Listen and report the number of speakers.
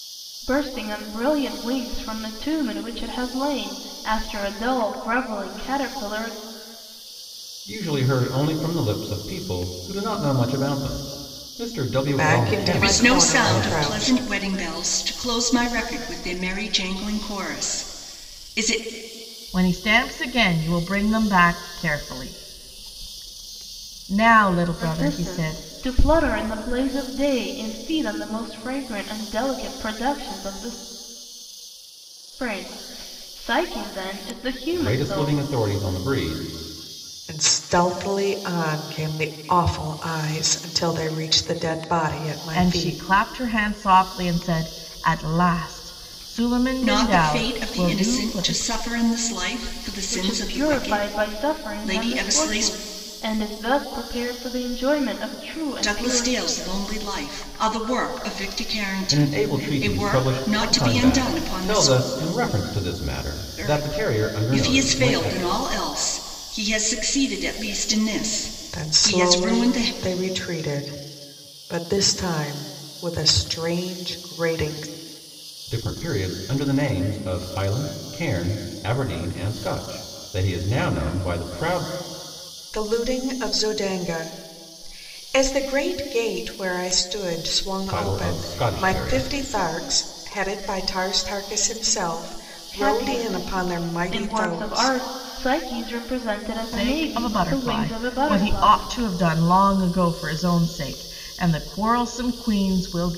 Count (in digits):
5